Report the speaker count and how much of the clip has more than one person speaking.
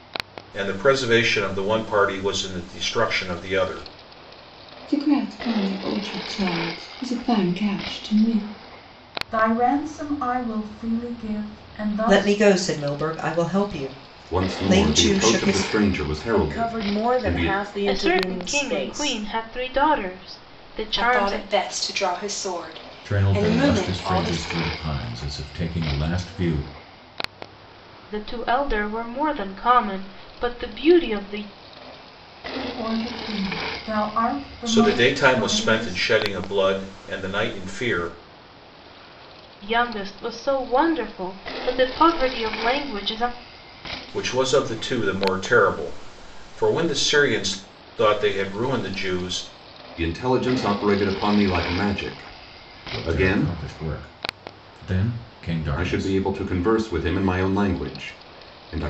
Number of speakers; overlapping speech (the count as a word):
nine, about 15%